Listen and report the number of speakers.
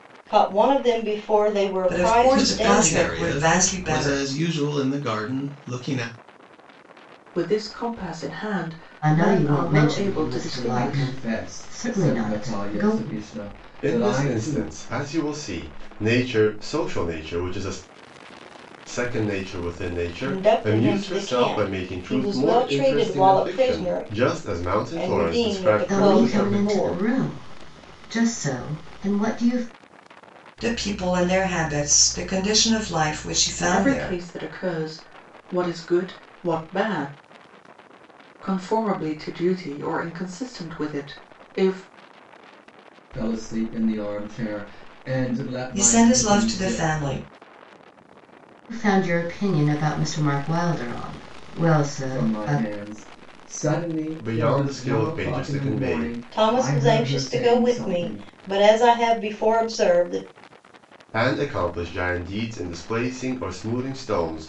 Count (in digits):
7